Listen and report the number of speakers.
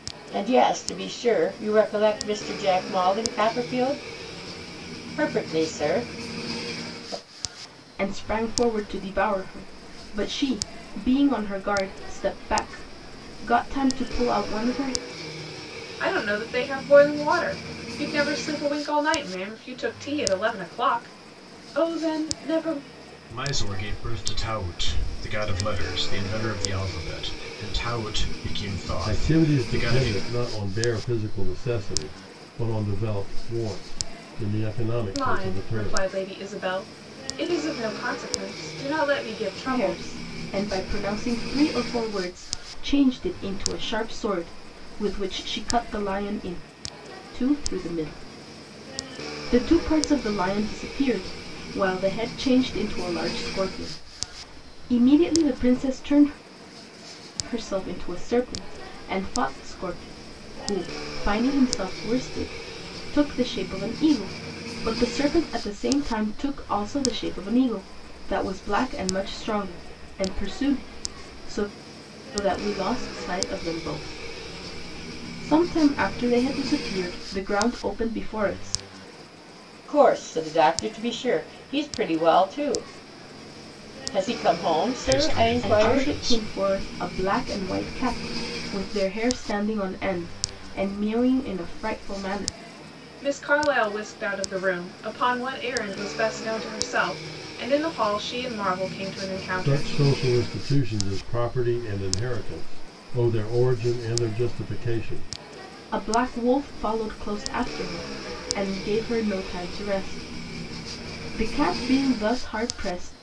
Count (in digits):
5